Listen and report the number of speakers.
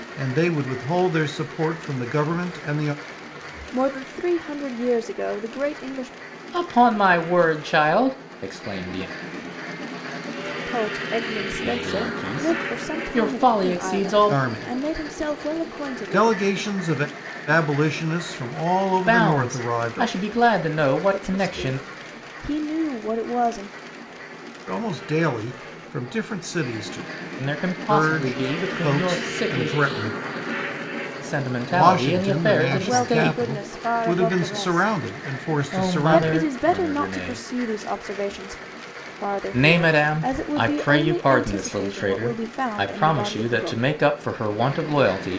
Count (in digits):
3